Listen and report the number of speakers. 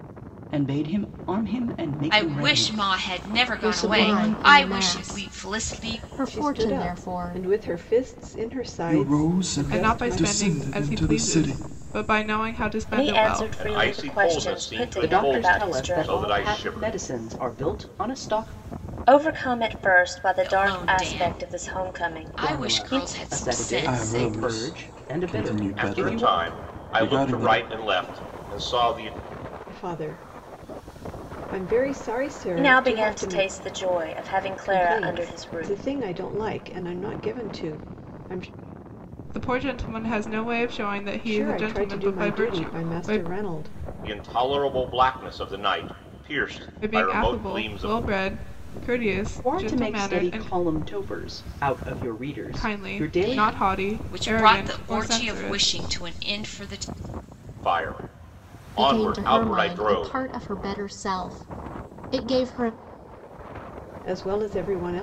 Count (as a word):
nine